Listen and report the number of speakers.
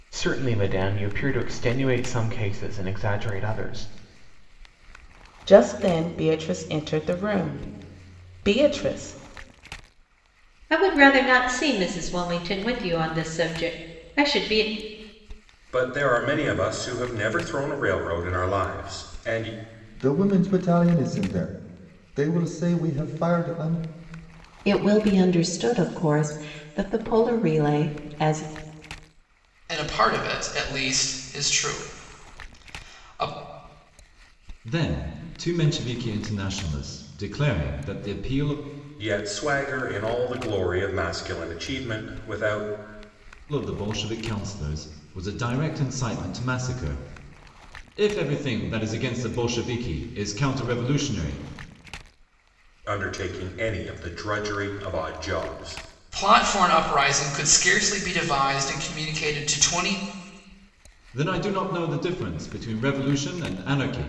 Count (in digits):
8